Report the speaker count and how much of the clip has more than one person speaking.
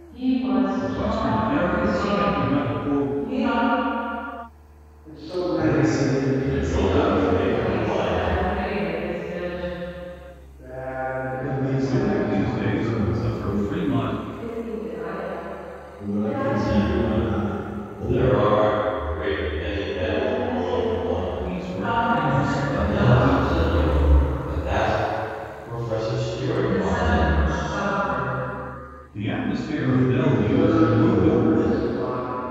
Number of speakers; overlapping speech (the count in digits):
7, about 54%